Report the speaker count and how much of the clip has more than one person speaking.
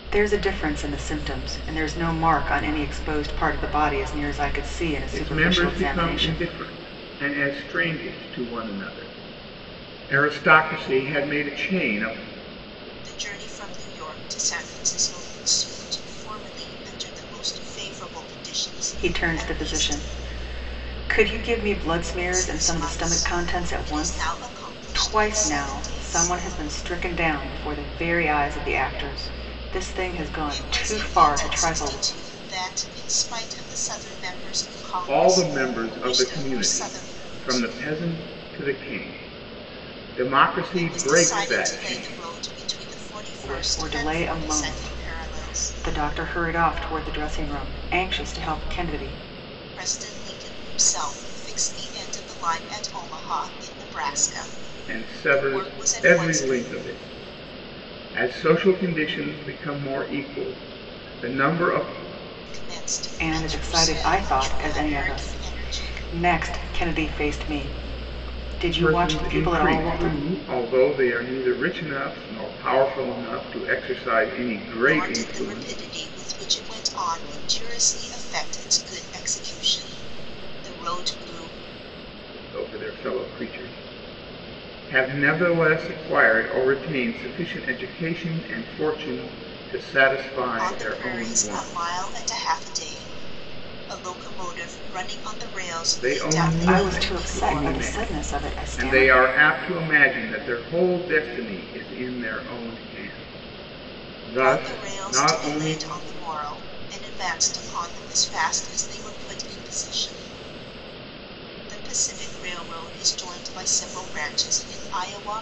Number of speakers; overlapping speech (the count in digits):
3, about 23%